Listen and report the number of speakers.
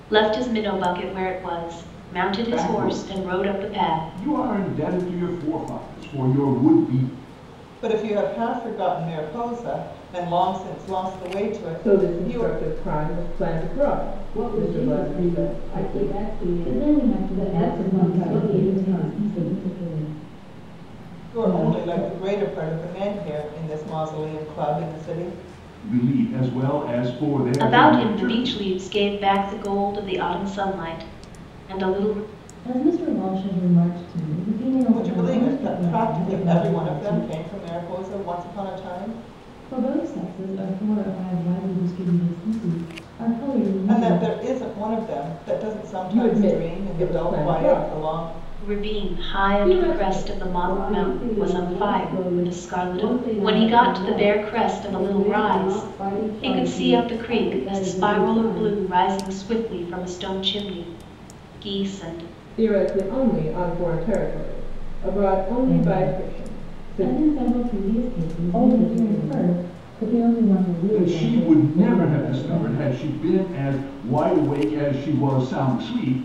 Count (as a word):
seven